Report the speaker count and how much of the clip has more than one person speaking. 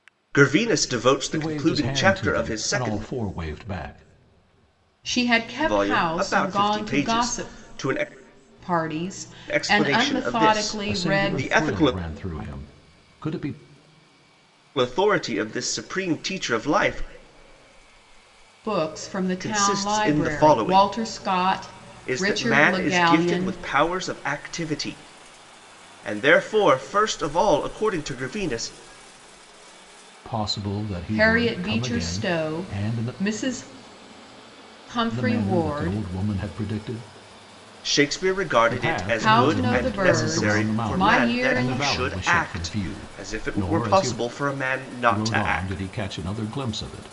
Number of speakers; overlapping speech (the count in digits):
3, about 40%